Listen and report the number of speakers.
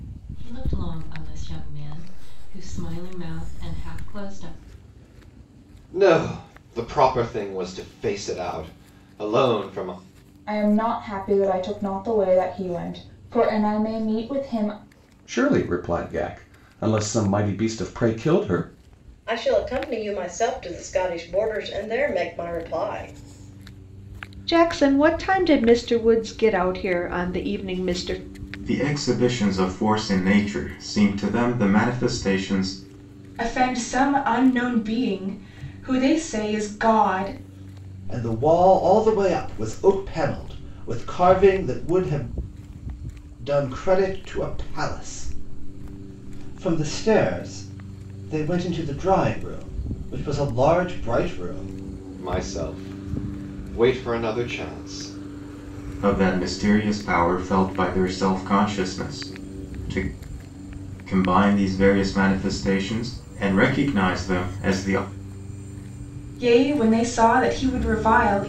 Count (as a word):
nine